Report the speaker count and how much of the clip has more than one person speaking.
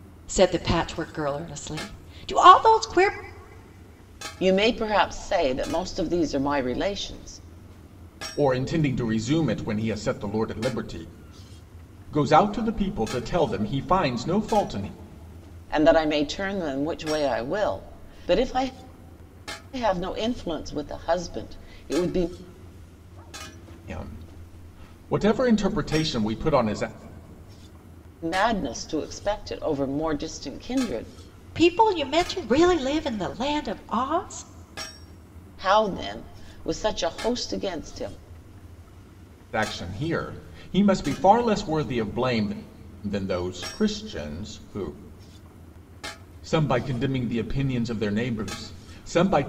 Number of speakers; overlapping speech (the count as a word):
three, no overlap